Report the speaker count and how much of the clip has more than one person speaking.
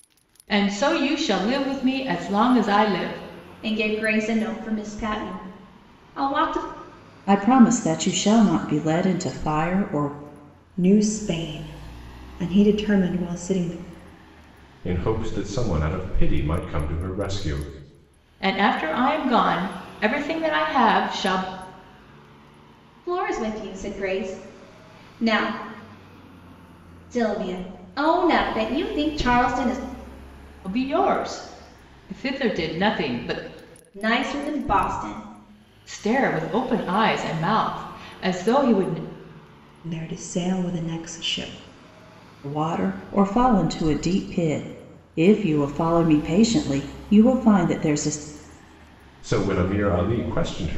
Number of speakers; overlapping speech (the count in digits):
5, no overlap